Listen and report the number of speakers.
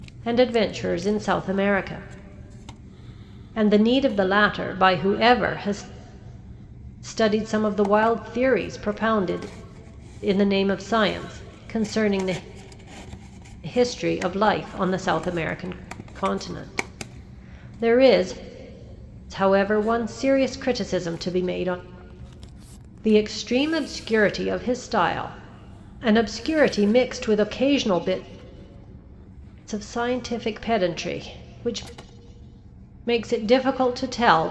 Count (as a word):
one